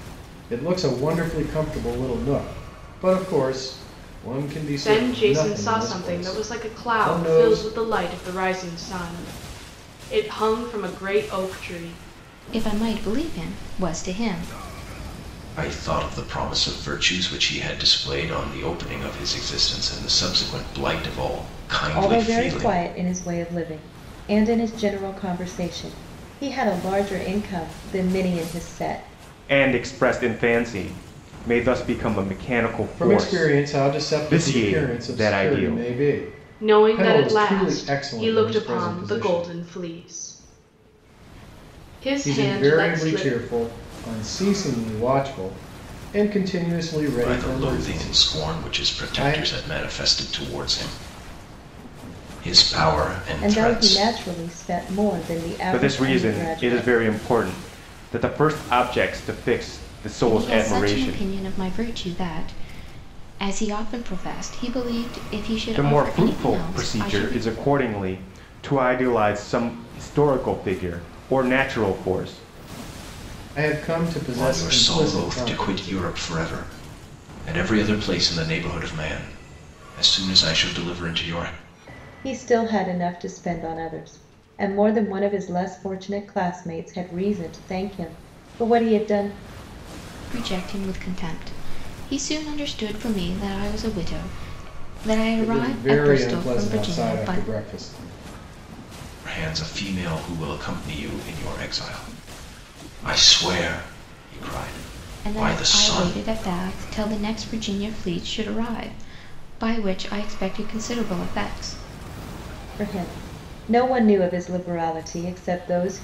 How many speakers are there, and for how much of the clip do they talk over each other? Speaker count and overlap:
6, about 20%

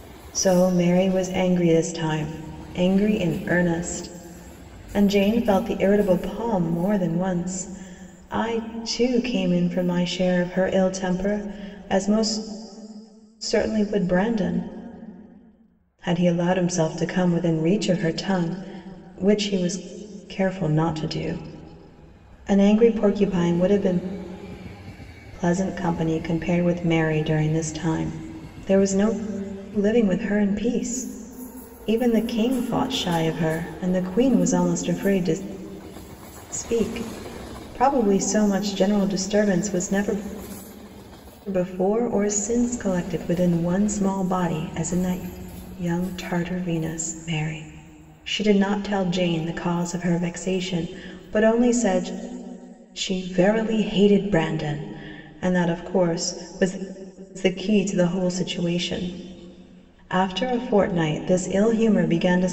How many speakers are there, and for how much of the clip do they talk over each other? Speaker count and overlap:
1, no overlap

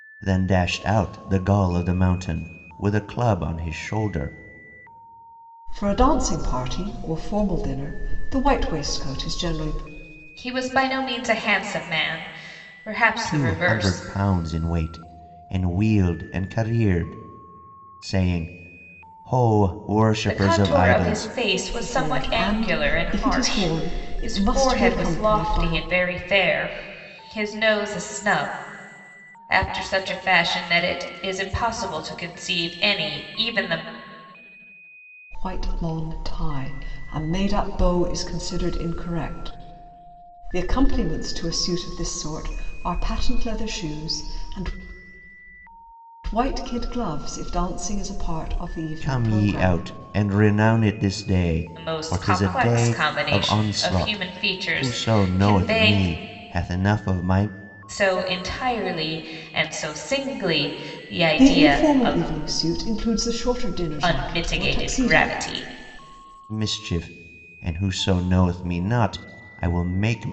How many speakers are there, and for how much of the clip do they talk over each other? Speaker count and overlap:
3, about 19%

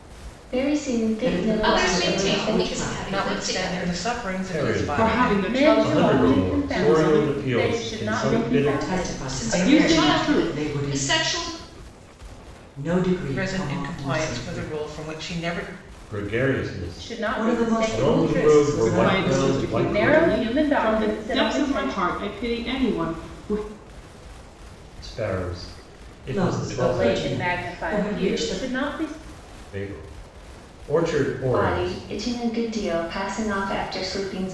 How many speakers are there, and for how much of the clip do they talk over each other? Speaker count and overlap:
7, about 54%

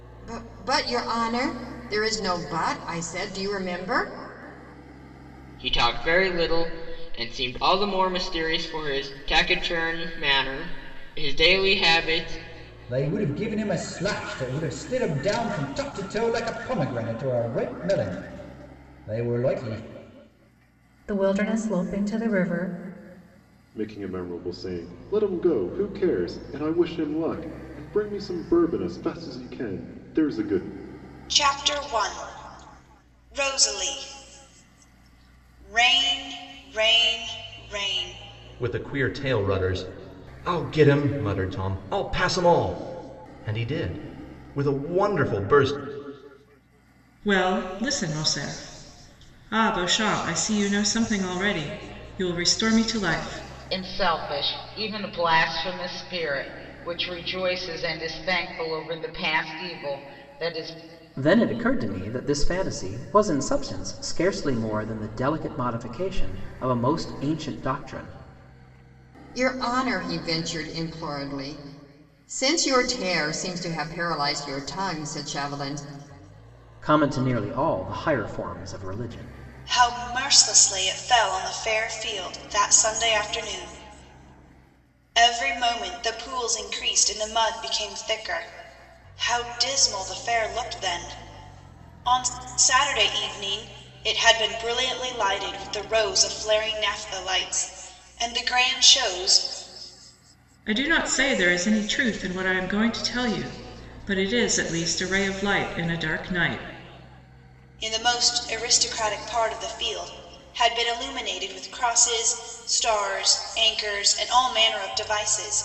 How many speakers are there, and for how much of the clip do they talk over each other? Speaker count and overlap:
10, no overlap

